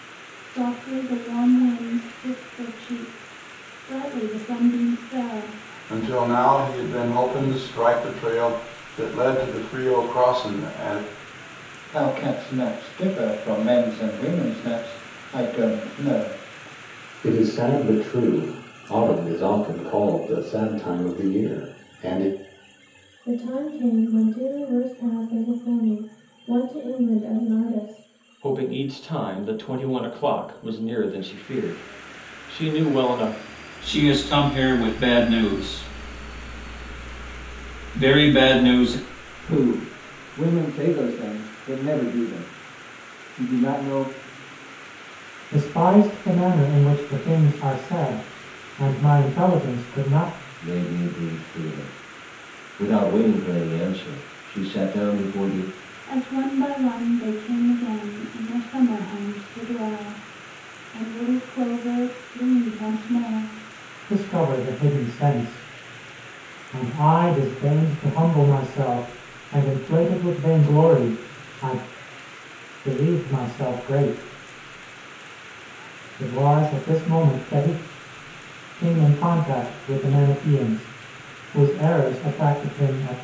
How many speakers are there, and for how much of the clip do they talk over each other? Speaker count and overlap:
10, no overlap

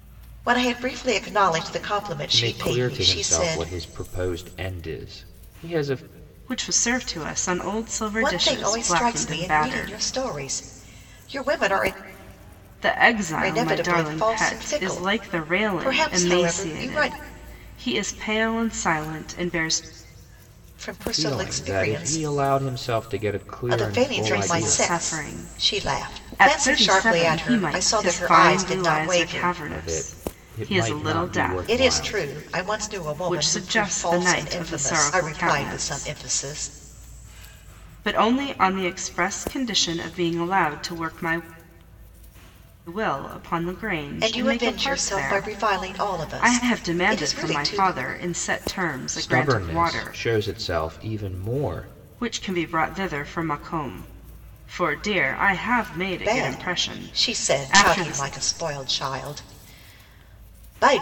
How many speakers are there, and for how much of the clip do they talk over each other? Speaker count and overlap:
3, about 43%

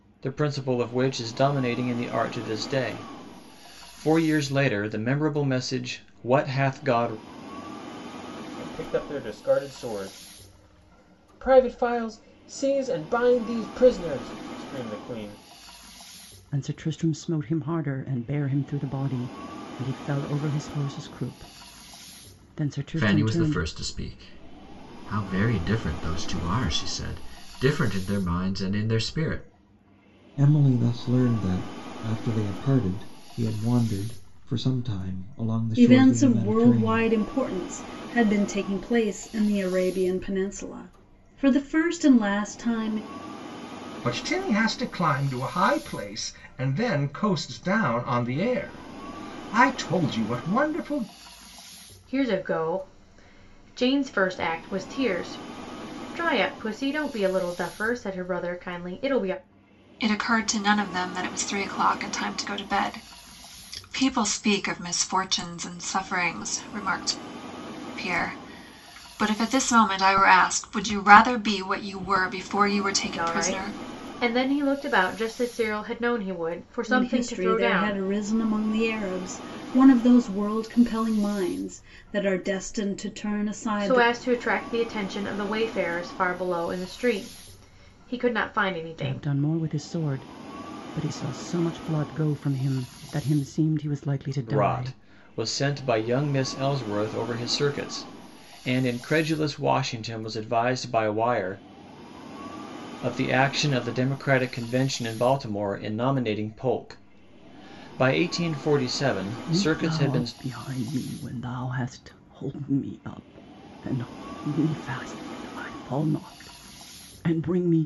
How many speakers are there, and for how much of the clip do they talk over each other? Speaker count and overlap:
9, about 5%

